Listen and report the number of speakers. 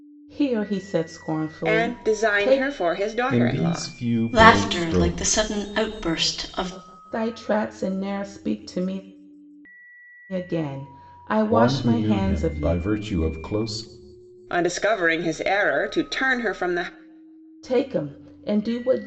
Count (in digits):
4